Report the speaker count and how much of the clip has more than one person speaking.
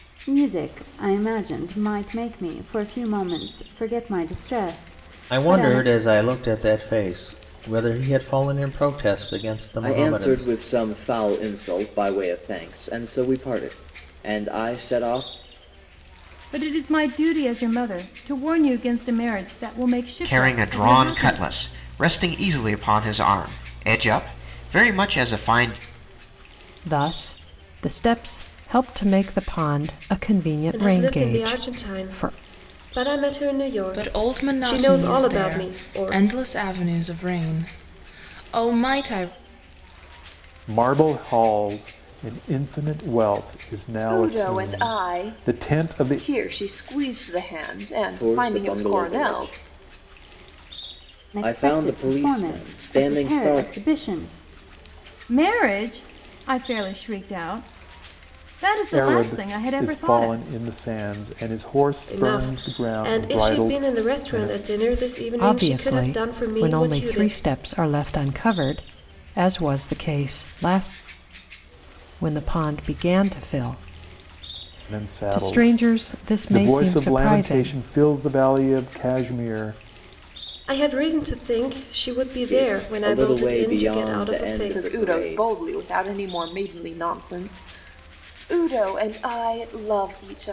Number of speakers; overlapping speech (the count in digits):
10, about 28%